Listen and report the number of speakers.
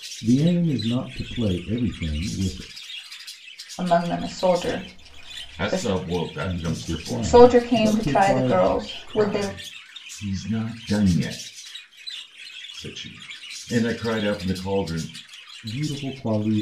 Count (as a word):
three